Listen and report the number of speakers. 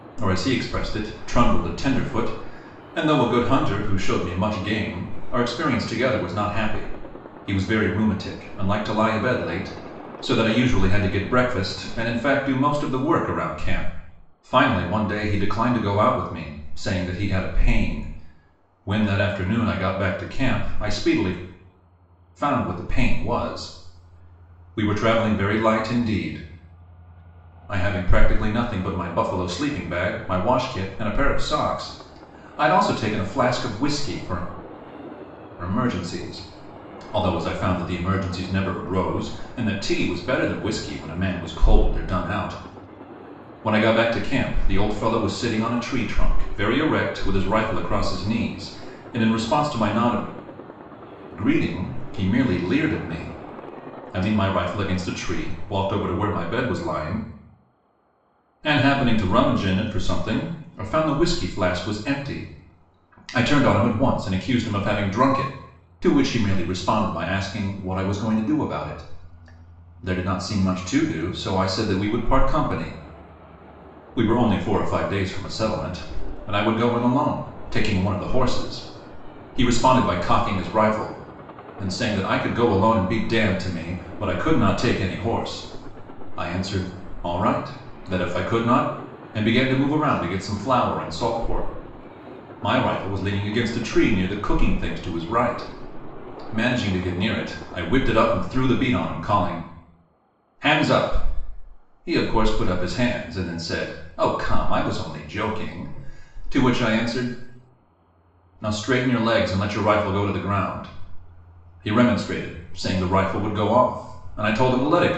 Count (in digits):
1